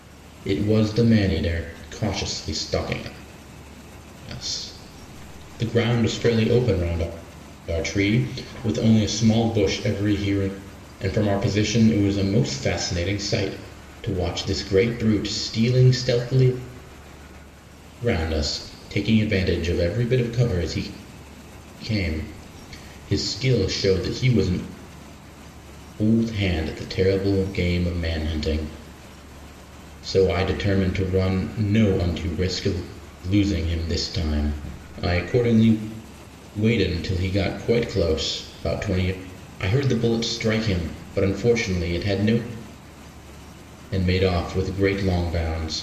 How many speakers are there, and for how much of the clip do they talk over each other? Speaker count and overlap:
1, no overlap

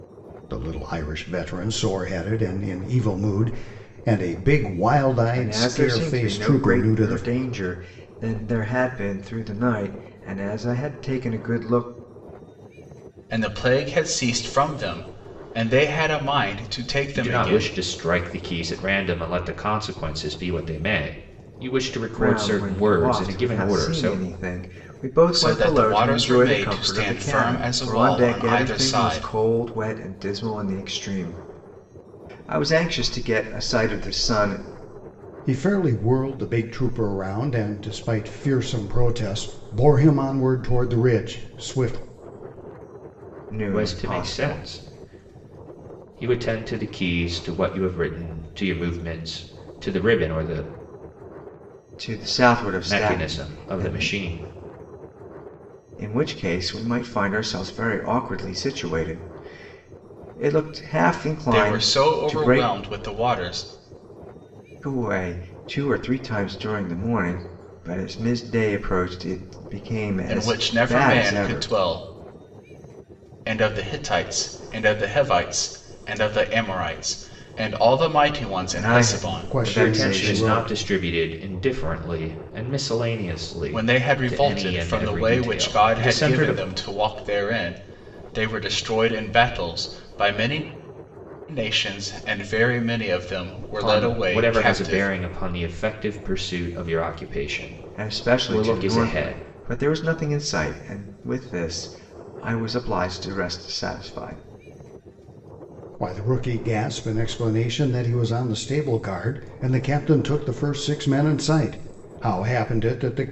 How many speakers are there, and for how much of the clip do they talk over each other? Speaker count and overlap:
4, about 19%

